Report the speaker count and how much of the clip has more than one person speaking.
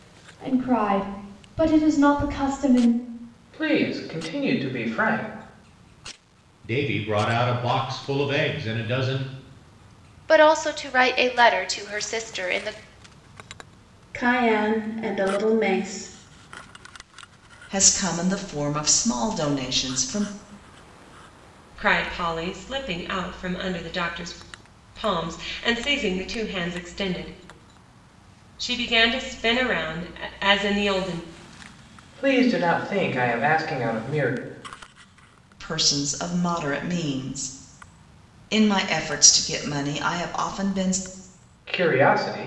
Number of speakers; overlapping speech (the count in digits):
7, no overlap